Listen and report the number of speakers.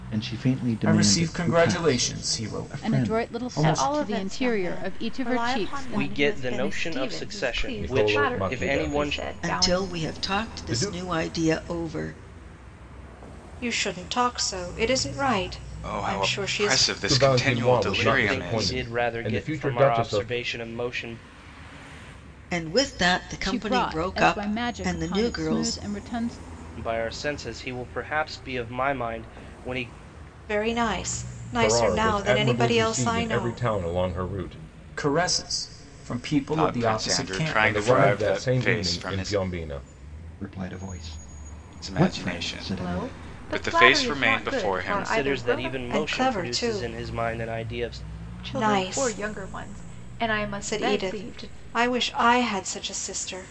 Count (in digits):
10